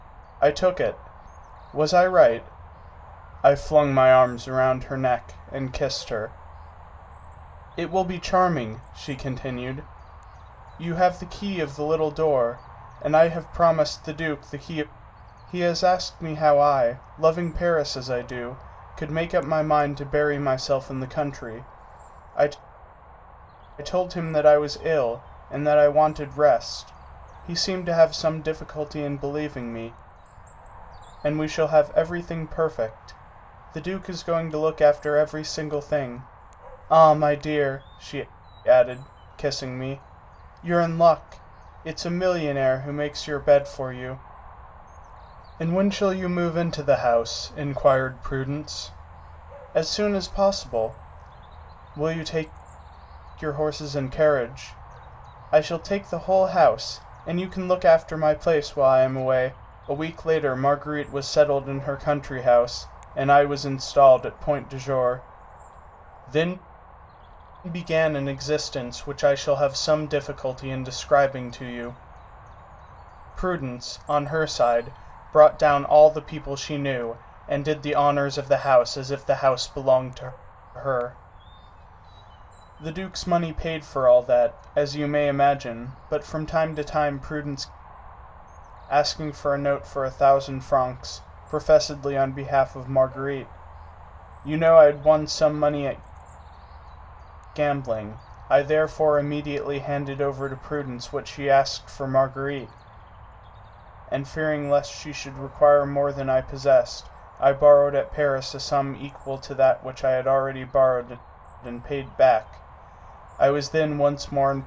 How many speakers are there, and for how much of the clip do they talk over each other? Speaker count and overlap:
1, no overlap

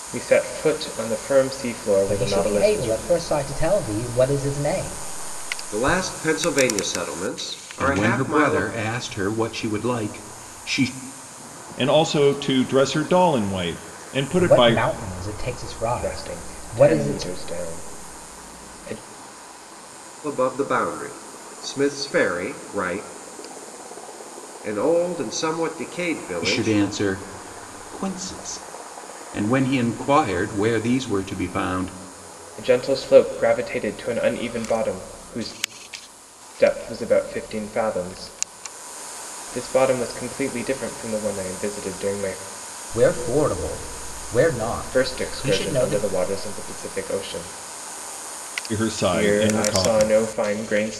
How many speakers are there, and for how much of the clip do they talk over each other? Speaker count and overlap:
5, about 13%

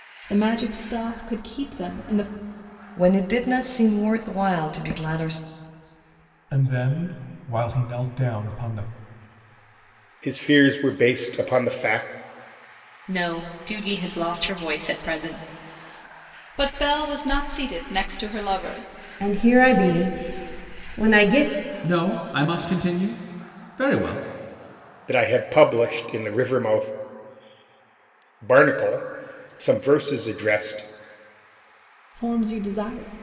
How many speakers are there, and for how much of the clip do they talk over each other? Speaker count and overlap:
8, no overlap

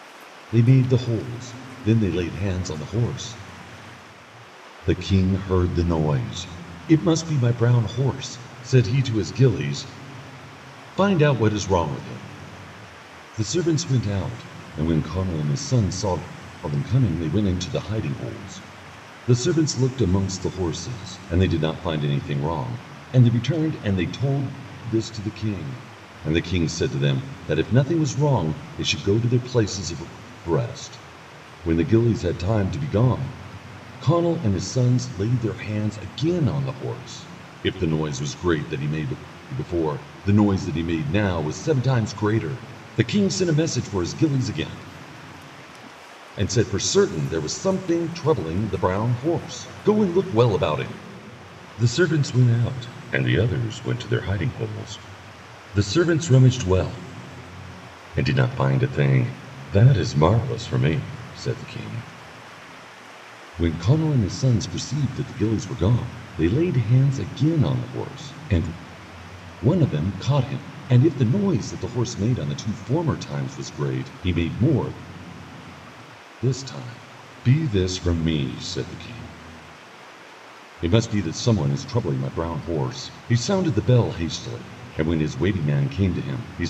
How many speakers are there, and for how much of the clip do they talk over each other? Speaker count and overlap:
1, no overlap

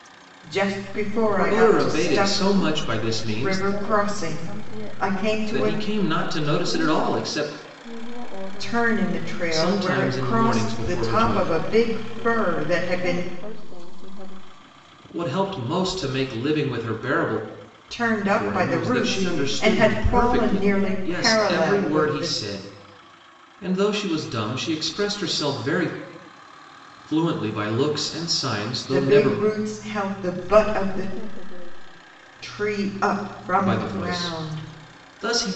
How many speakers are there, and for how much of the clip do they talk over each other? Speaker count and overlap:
3, about 49%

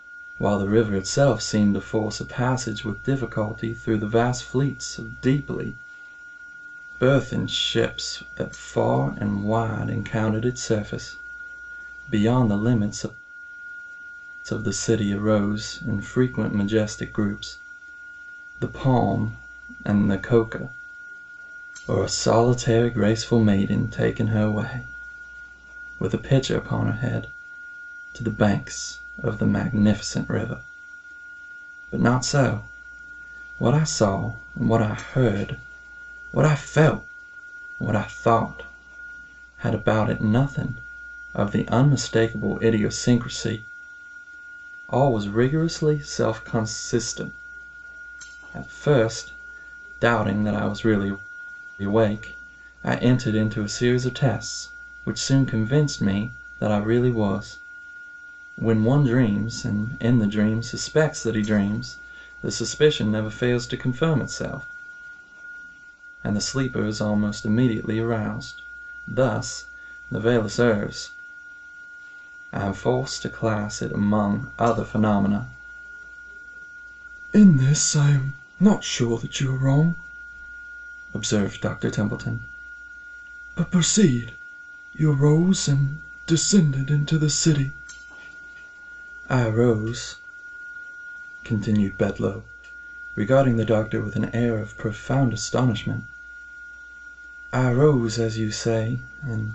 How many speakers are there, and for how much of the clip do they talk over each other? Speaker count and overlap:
1, no overlap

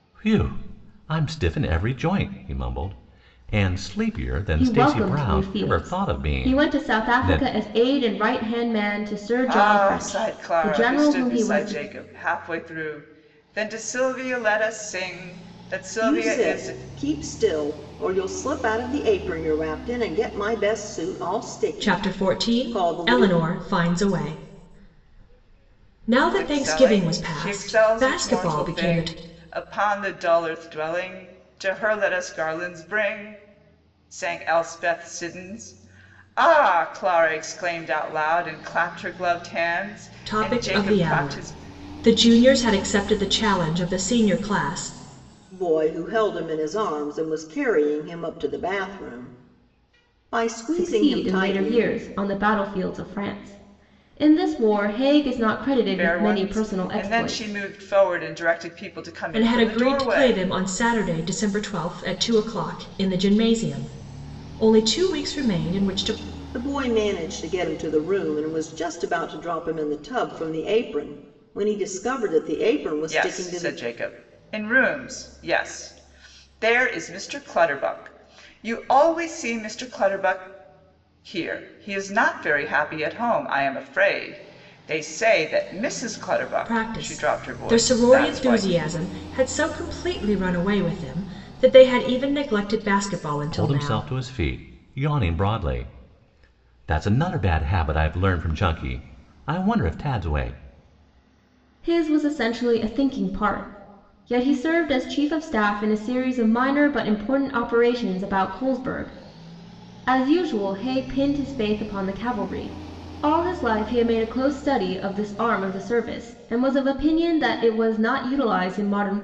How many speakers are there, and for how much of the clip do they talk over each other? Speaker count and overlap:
5, about 16%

